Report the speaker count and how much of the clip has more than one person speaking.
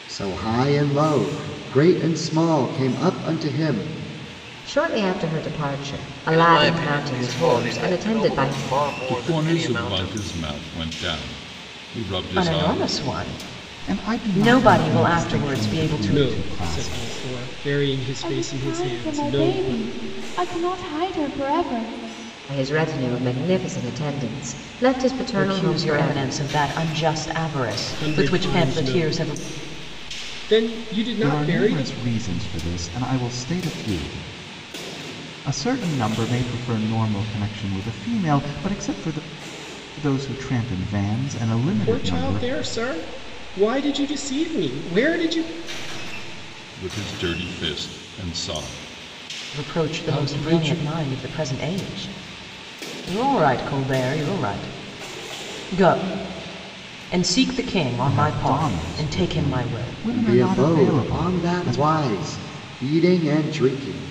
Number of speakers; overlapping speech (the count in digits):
8, about 29%